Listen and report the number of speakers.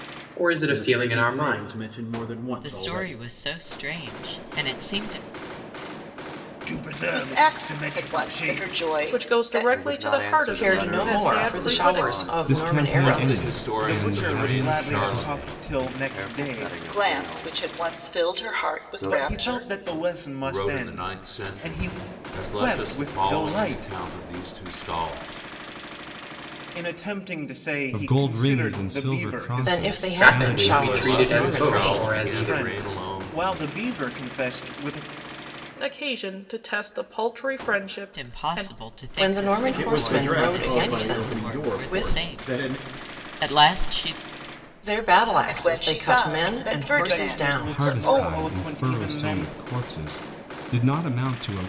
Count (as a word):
ten